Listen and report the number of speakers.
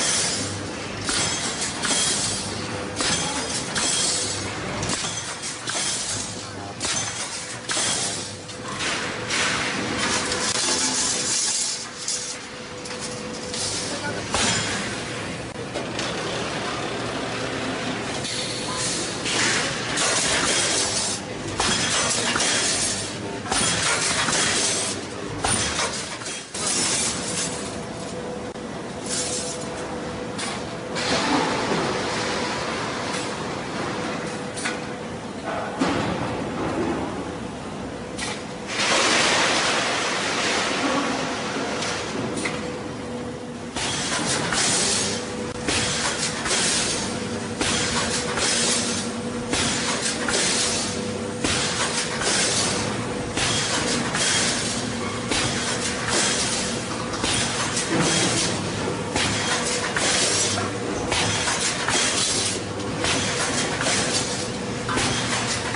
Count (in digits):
0